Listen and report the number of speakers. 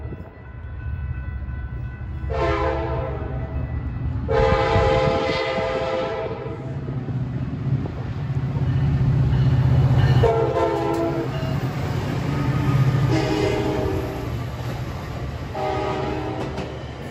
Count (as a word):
zero